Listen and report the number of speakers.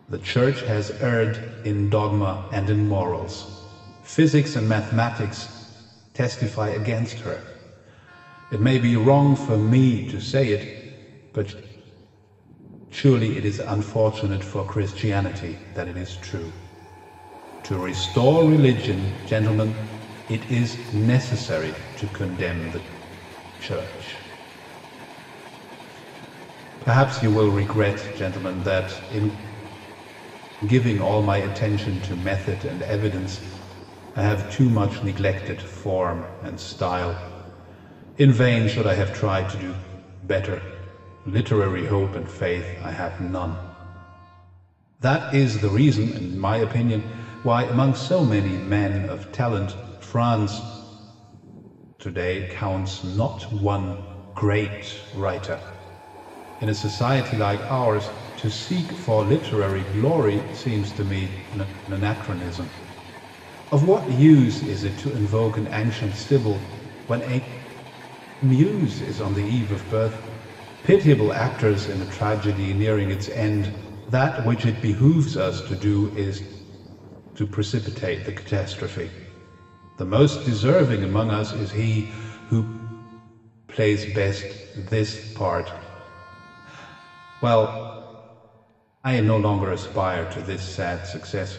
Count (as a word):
one